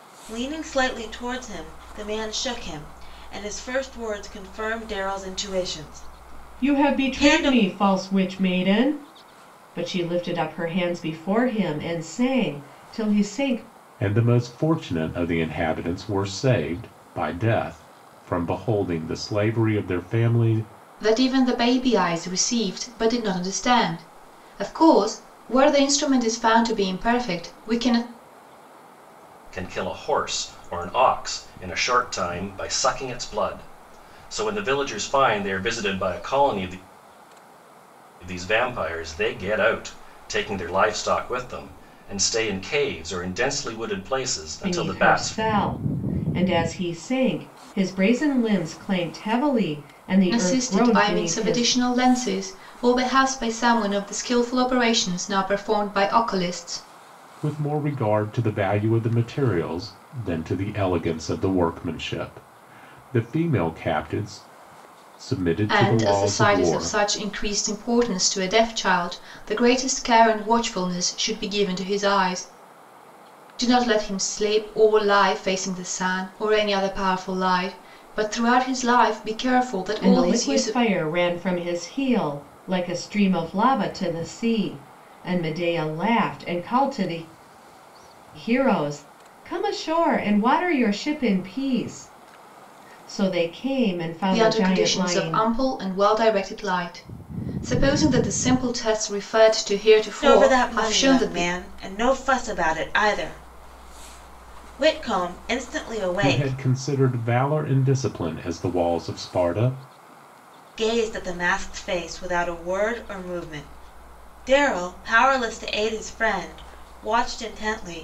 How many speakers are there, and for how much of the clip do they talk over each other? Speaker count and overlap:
5, about 7%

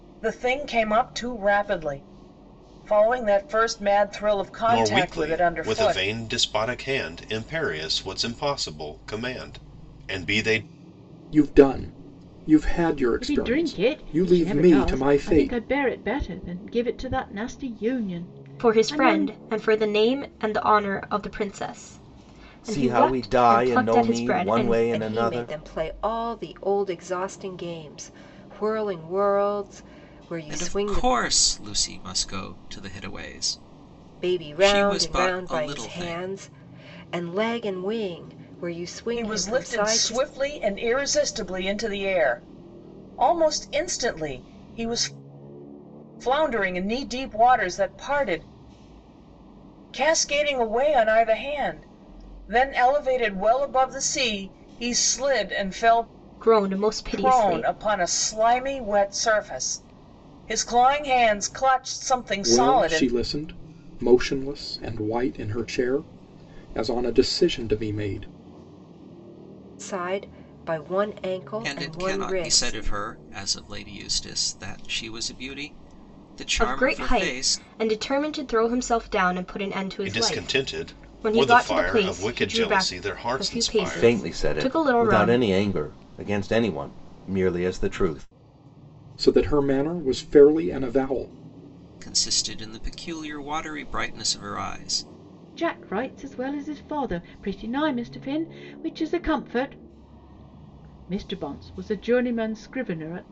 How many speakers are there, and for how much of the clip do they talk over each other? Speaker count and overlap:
8, about 20%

